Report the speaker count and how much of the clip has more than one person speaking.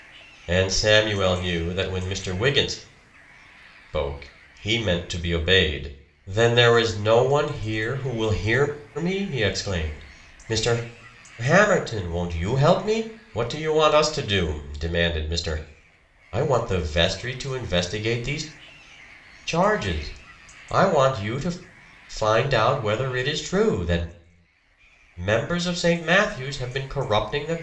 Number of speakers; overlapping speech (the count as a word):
one, no overlap